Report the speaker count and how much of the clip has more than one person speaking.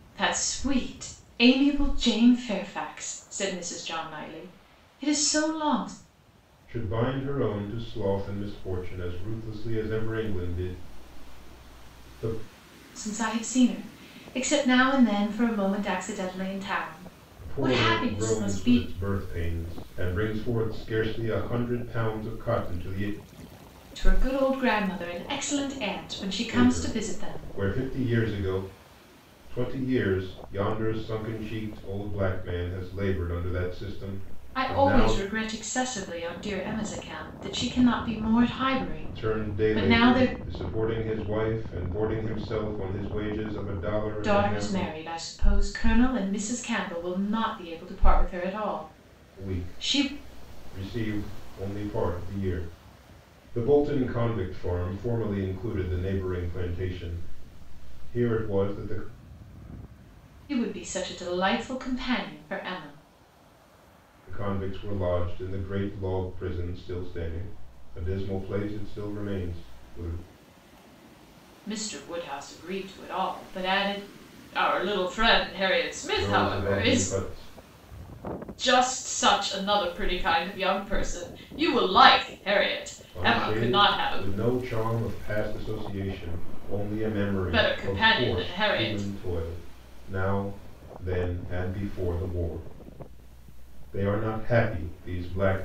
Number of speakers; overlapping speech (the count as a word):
two, about 10%